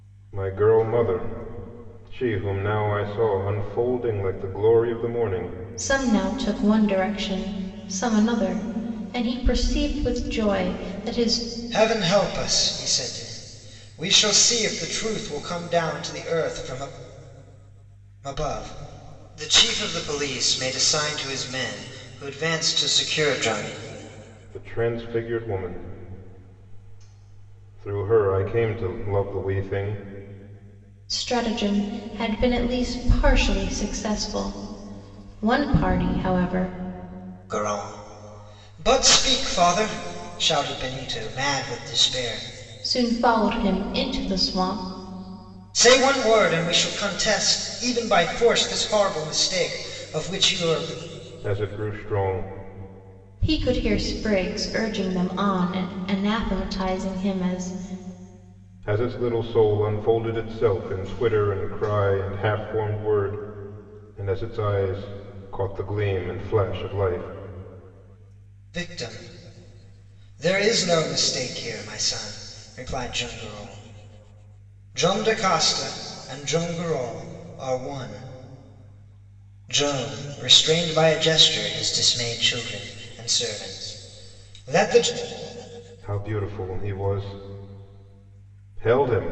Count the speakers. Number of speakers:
three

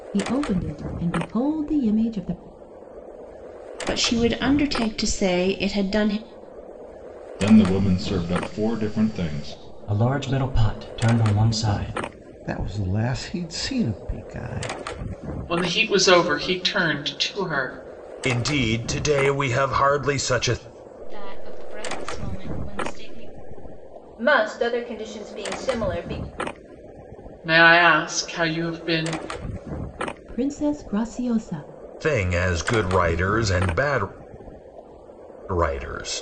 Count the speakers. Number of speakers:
nine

